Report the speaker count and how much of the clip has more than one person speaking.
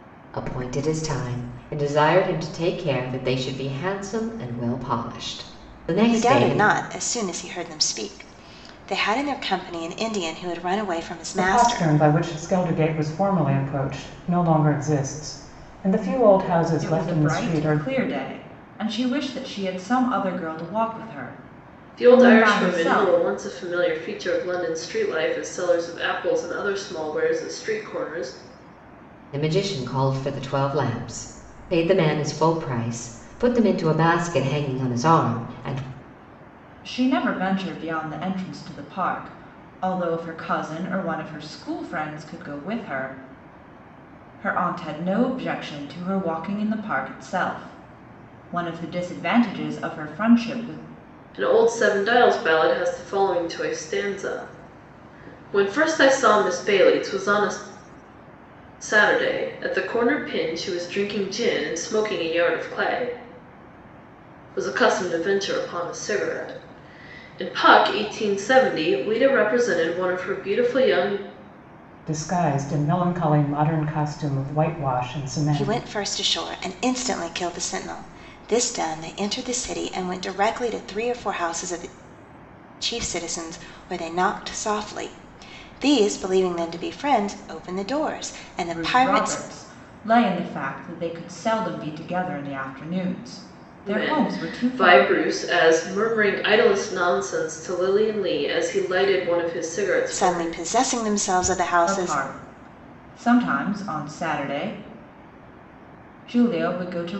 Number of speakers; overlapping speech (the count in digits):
5, about 6%